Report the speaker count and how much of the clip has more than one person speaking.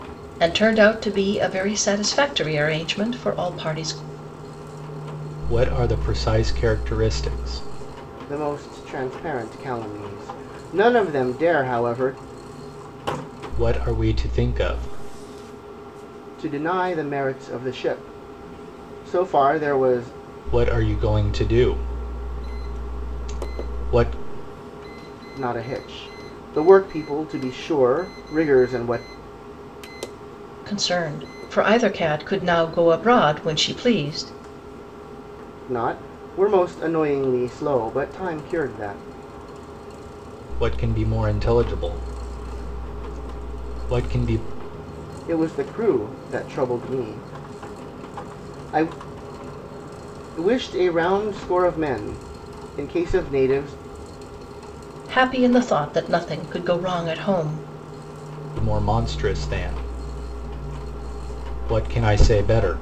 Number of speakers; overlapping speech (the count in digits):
3, no overlap